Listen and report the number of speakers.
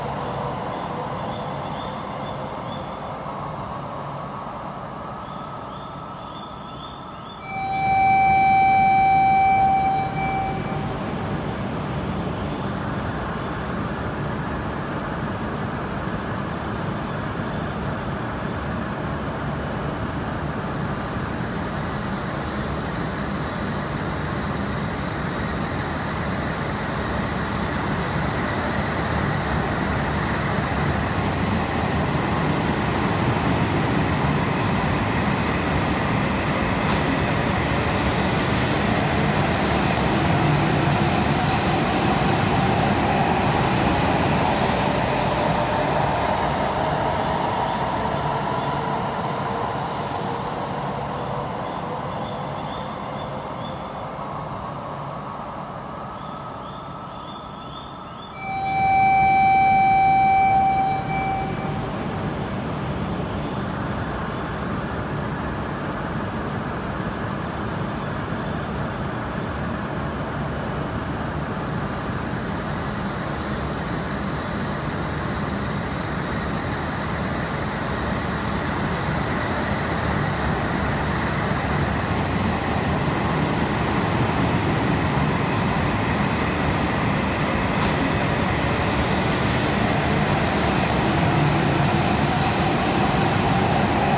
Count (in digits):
0